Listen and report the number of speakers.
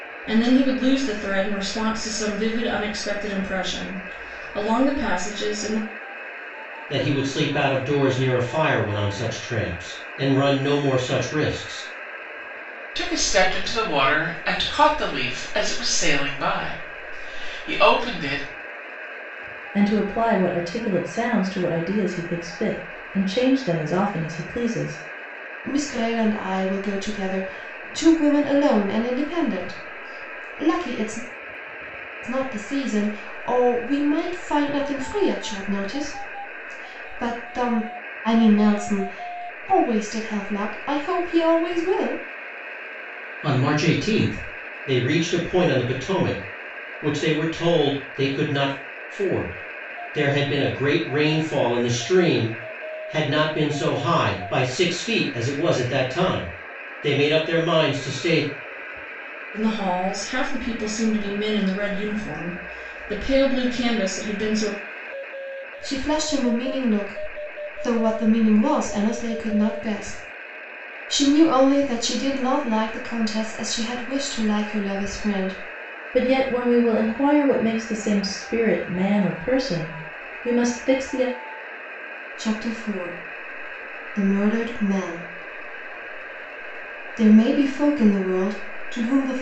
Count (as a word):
five